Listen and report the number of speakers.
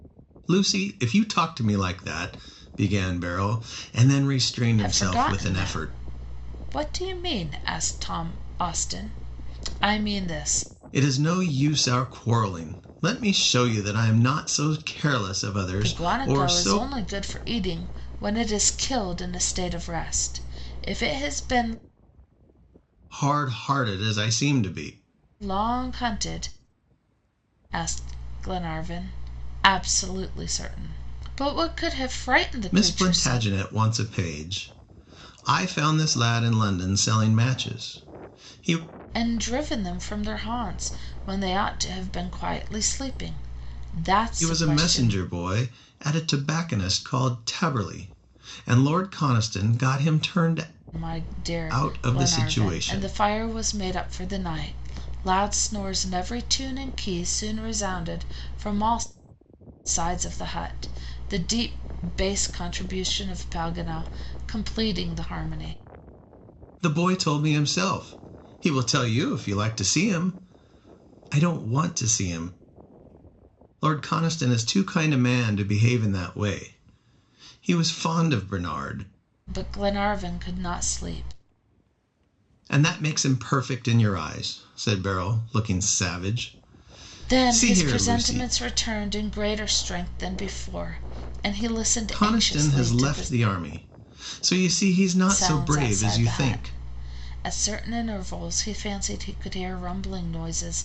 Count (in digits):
2